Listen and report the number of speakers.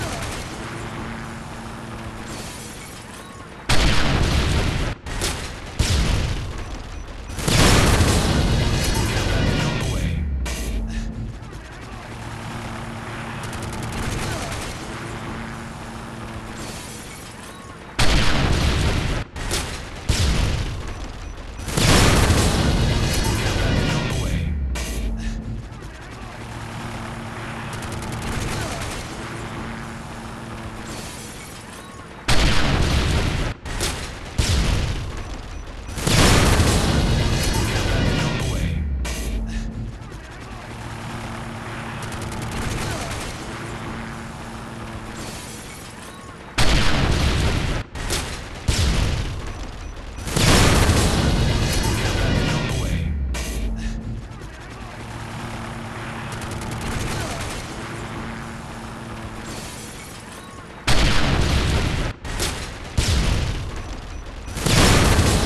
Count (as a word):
zero